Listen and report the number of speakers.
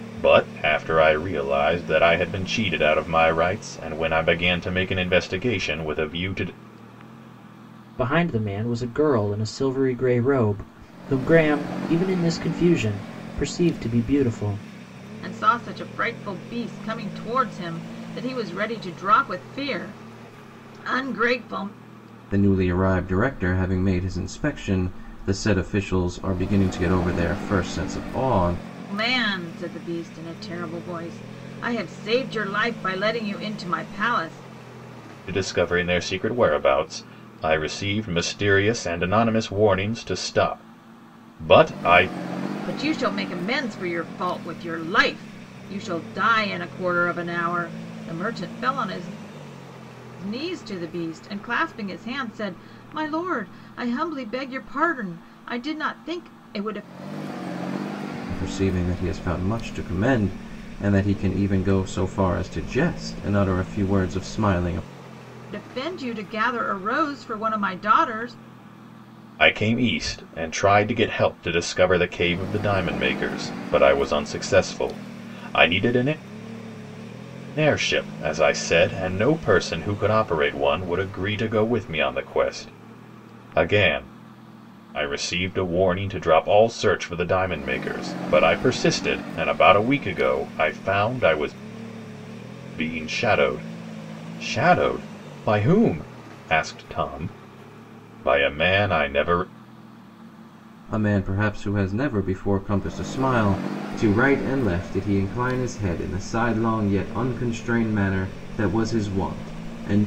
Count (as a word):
four